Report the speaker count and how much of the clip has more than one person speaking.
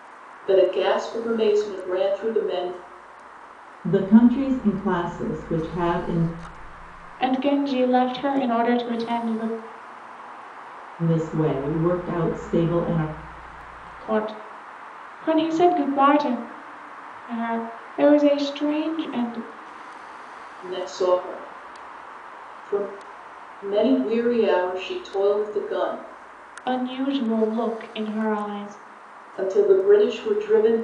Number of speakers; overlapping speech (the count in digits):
3, no overlap